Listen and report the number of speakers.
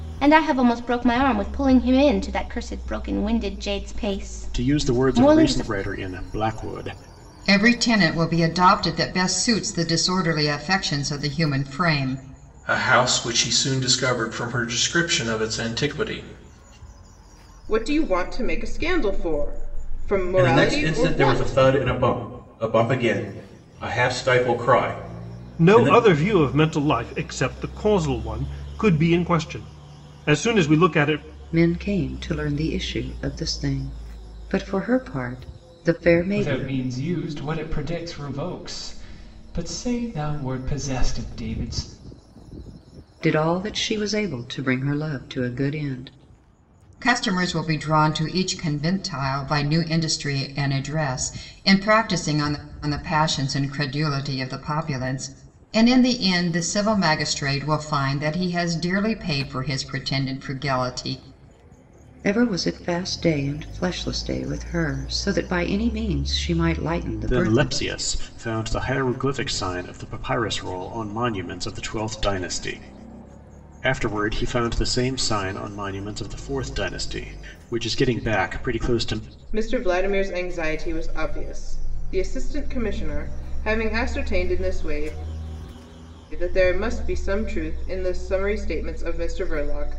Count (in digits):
9